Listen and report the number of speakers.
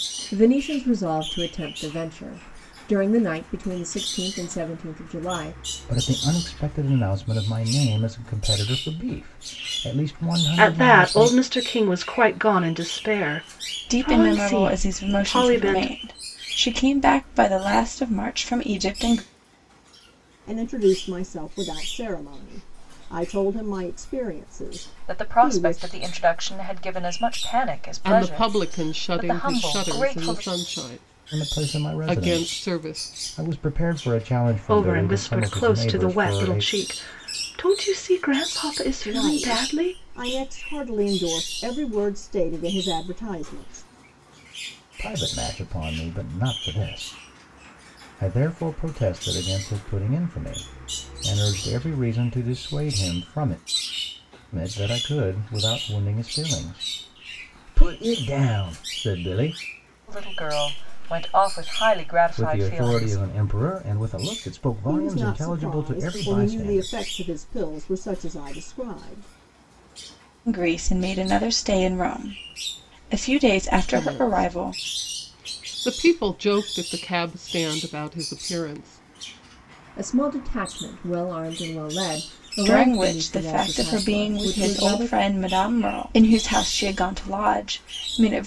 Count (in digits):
7